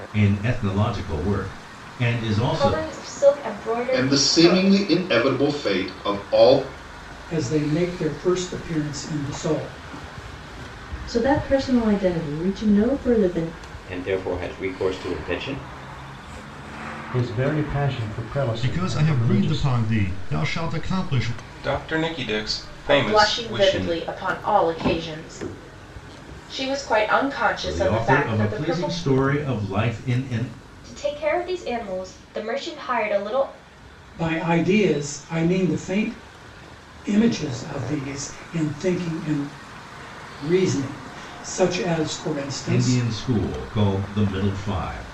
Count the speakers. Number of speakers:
10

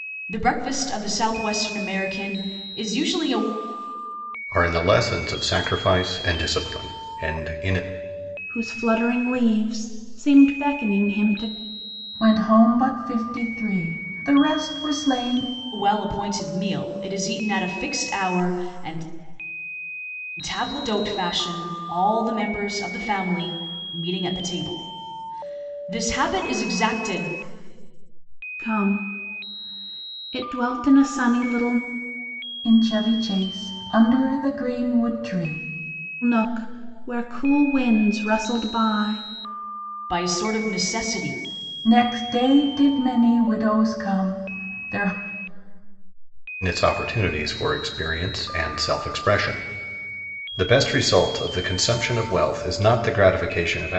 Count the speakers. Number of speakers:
4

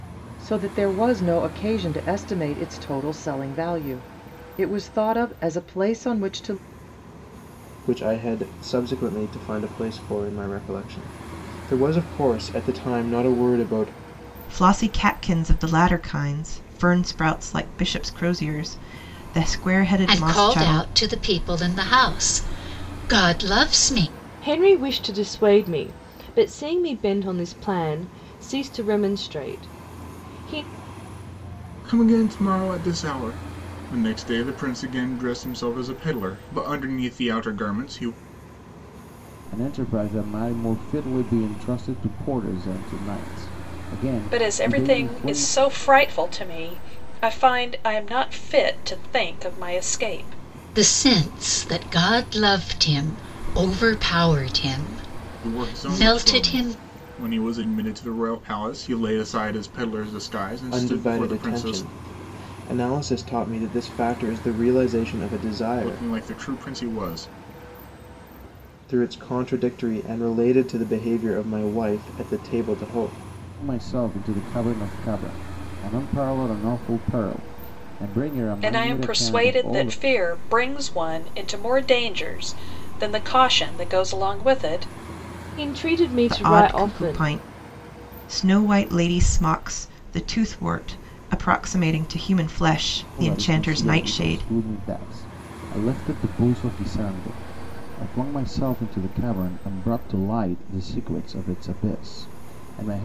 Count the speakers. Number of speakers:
8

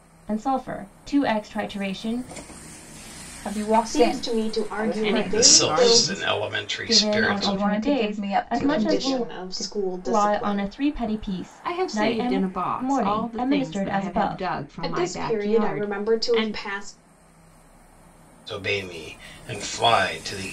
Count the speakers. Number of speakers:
5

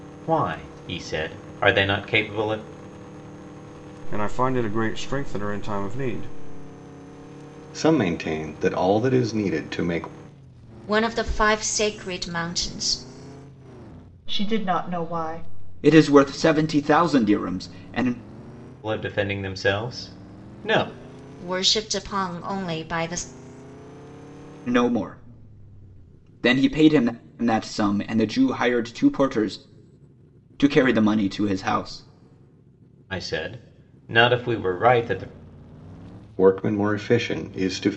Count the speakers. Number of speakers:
6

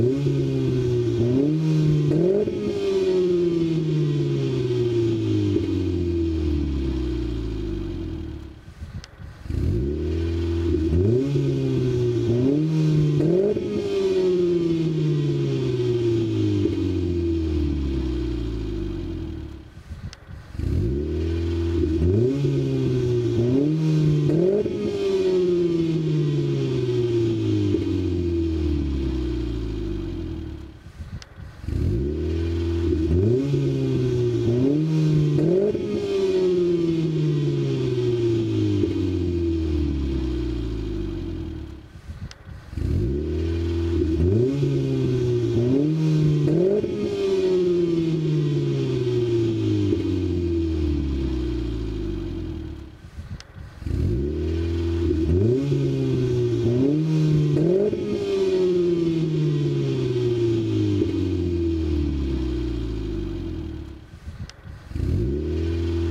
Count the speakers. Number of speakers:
0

